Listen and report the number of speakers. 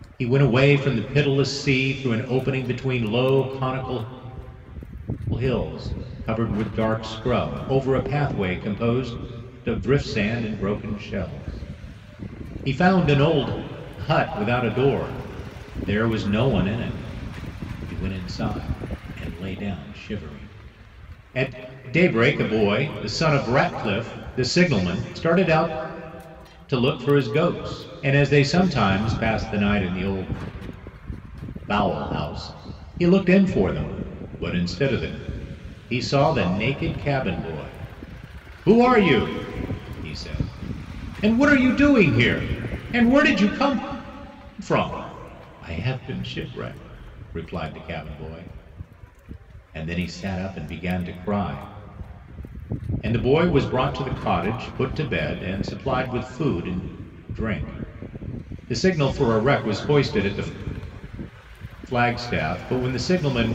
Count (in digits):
1